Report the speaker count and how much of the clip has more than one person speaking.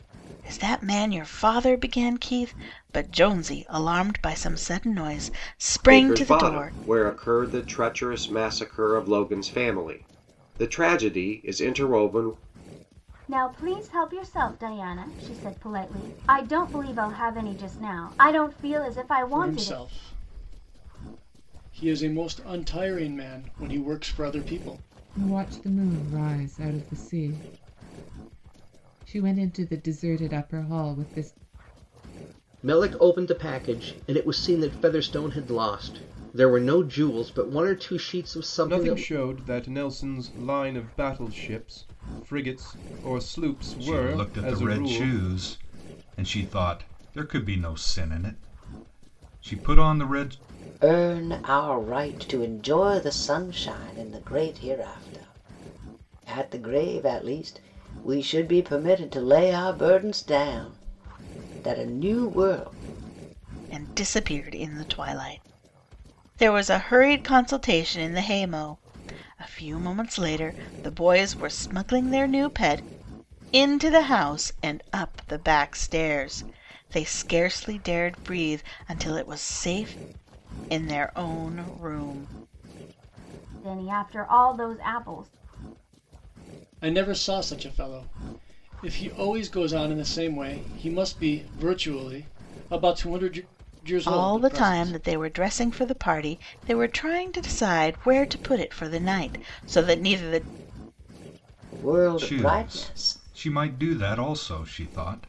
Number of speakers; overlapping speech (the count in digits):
9, about 5%